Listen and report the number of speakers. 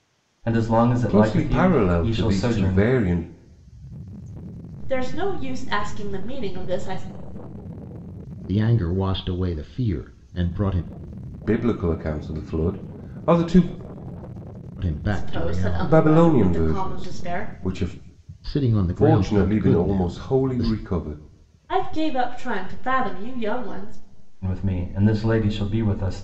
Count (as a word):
four